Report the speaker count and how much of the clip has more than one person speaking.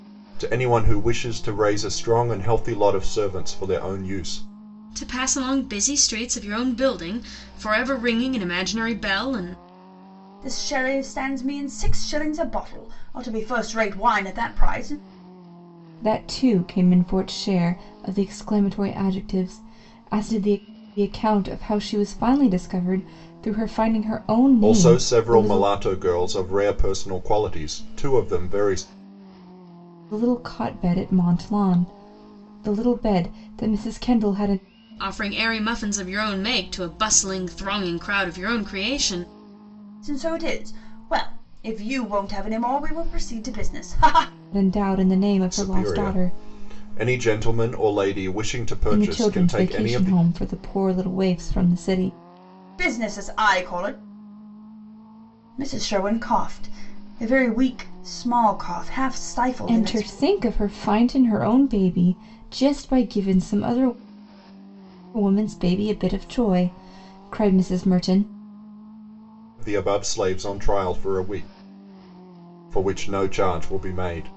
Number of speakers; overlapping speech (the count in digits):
4, about 5%